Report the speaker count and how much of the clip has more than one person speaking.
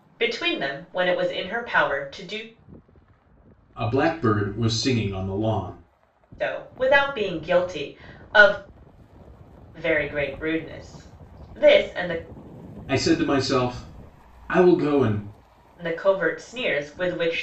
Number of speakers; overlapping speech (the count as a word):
two, no overlap